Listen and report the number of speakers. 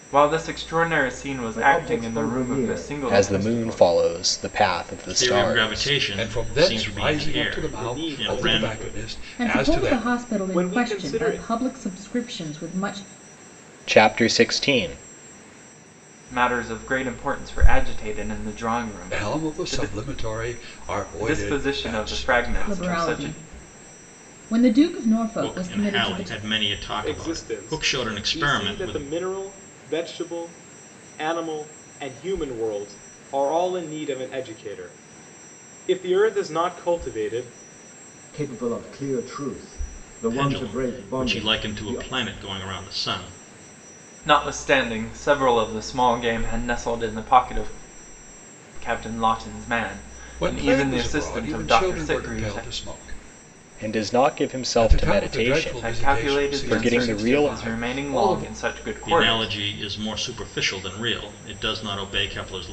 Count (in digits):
7